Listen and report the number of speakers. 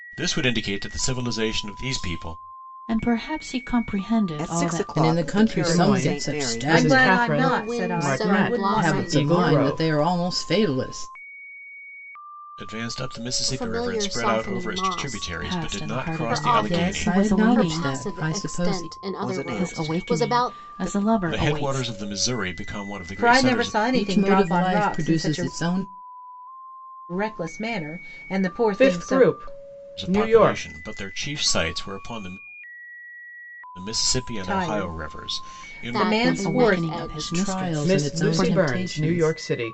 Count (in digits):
7